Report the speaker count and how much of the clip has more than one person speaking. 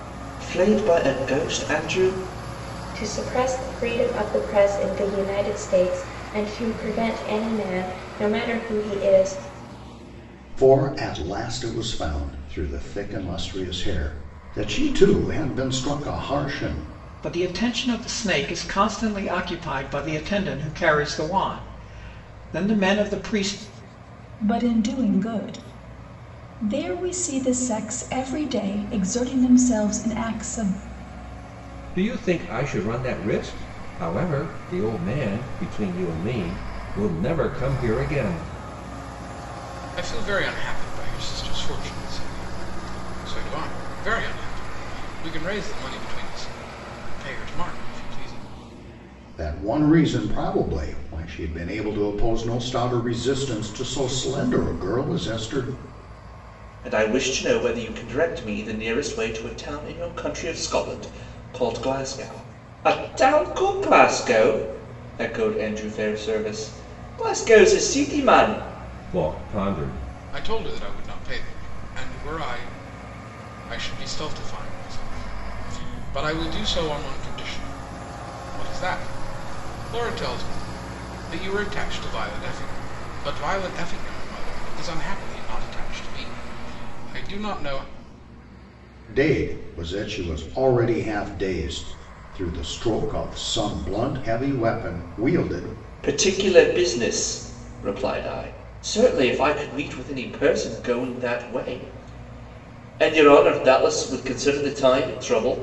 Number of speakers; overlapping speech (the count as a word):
seven, no overlap